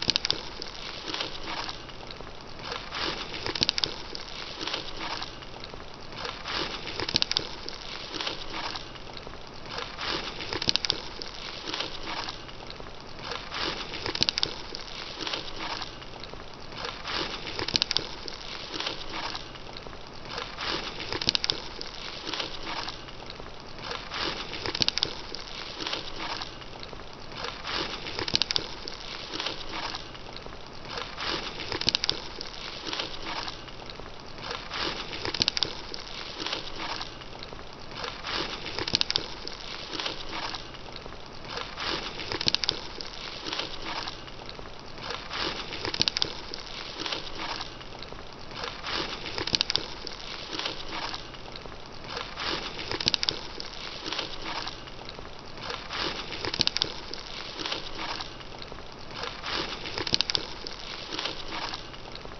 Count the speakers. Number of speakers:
0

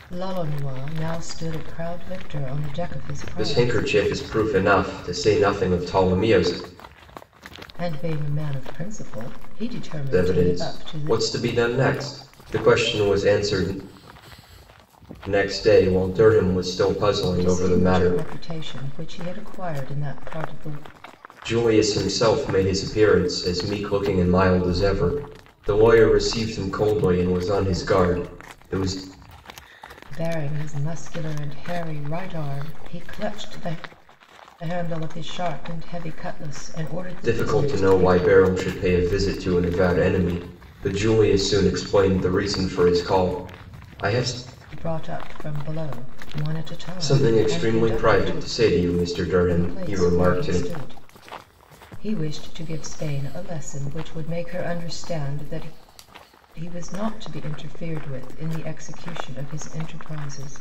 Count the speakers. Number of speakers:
2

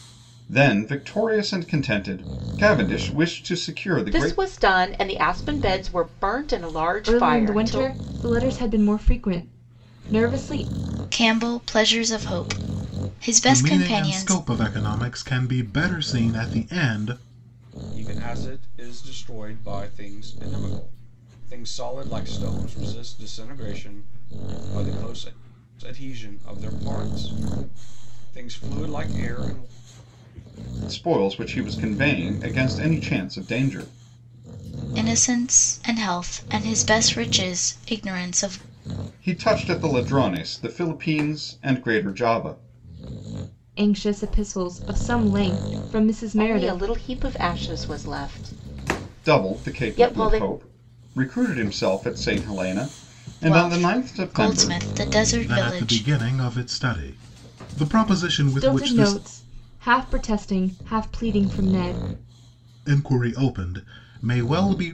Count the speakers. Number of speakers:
6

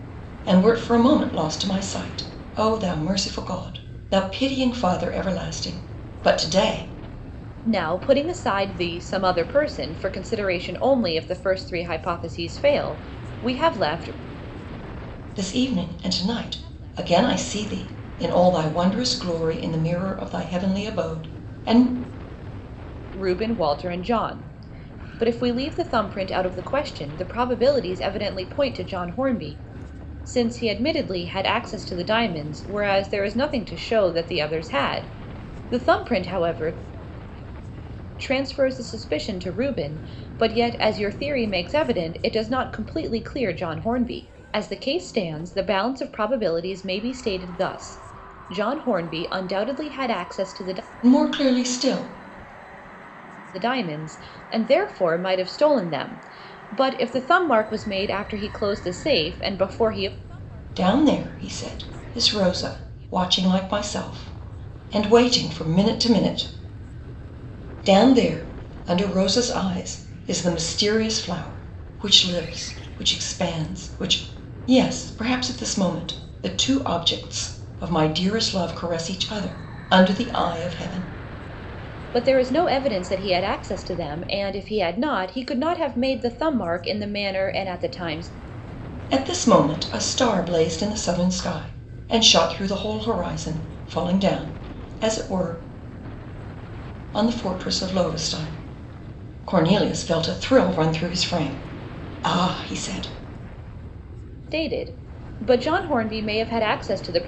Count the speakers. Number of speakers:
2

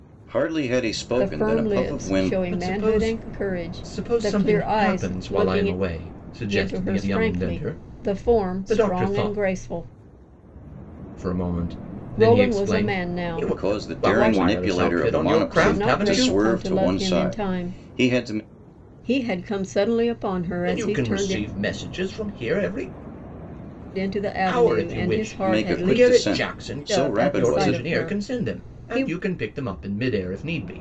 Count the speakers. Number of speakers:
3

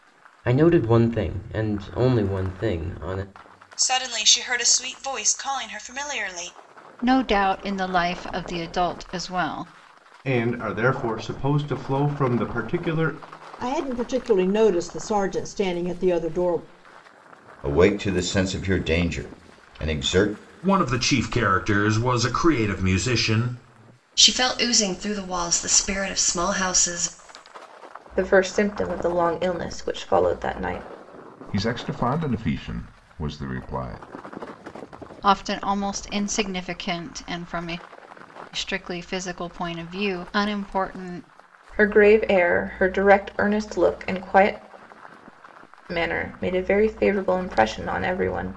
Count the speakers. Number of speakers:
10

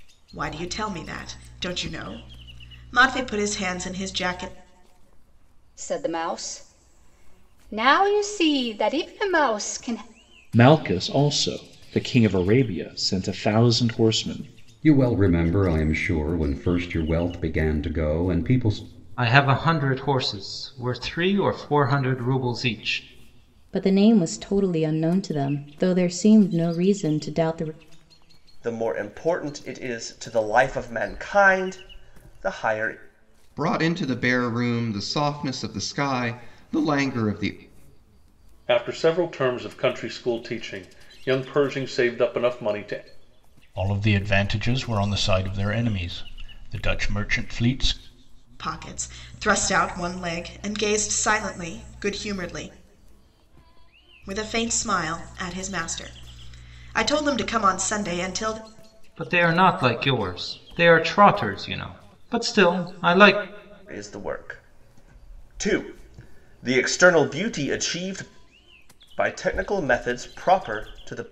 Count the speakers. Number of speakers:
10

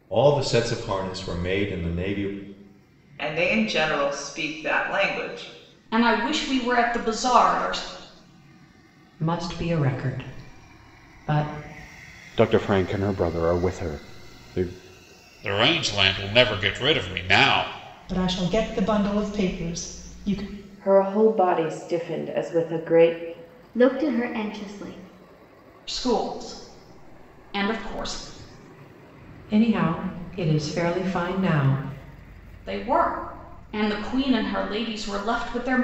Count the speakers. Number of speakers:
9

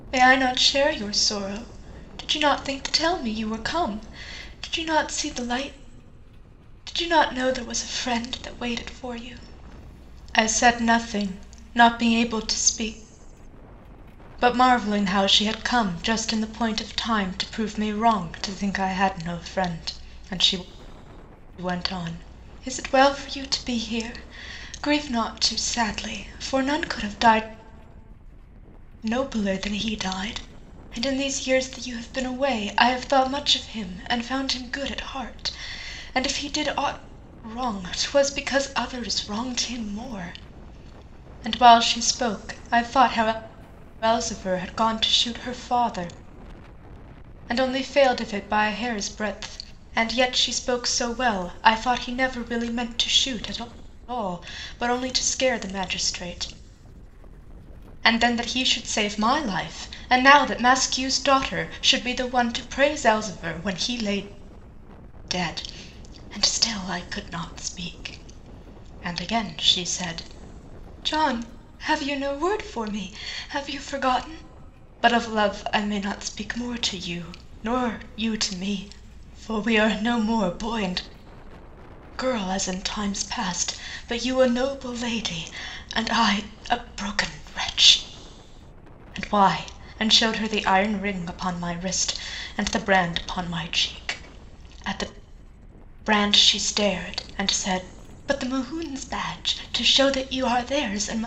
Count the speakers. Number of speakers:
1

